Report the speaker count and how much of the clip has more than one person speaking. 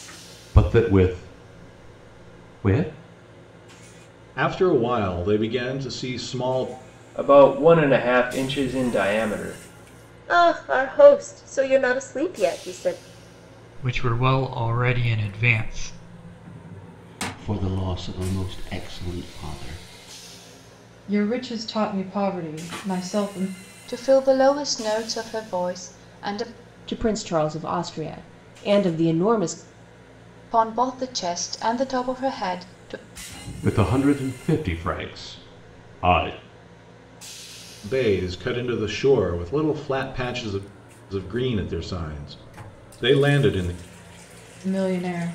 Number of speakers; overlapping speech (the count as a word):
nine, no overlap